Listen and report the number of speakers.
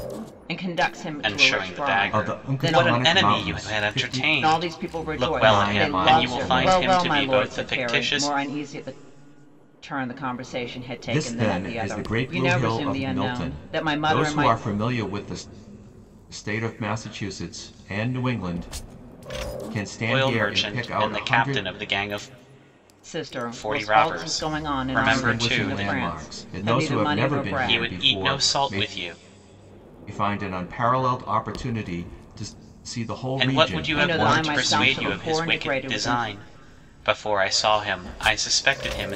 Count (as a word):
three